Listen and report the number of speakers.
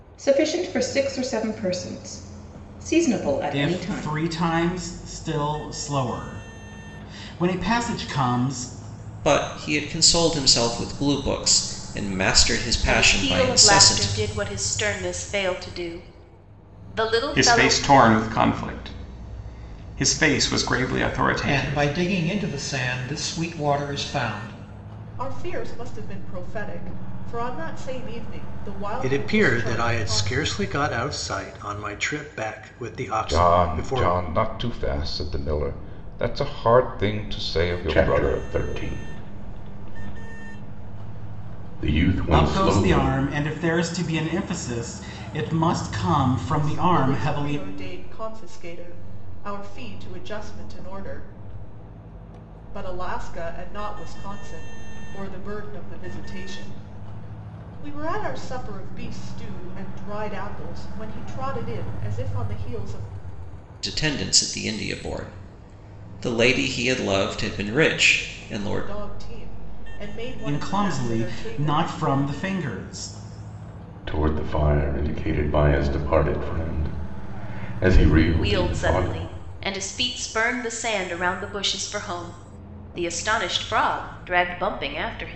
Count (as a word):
ten